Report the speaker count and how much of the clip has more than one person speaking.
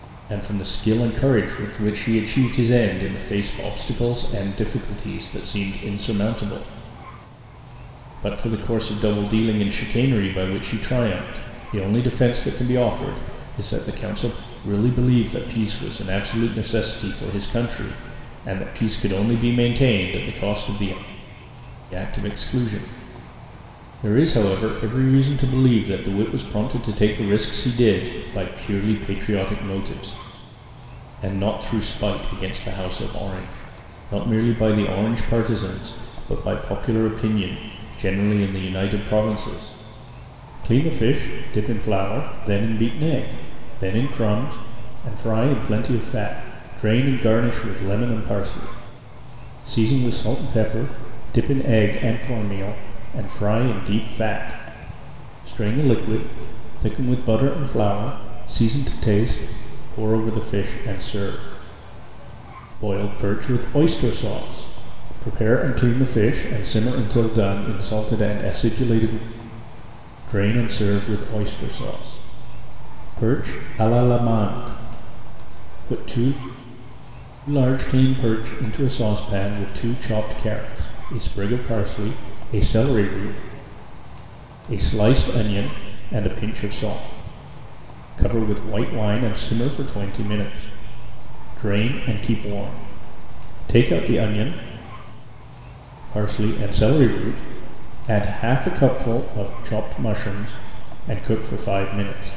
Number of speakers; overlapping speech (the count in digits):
1, no overlap